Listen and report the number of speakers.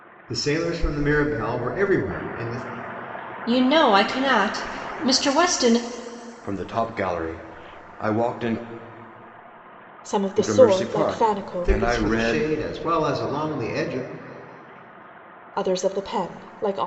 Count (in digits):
4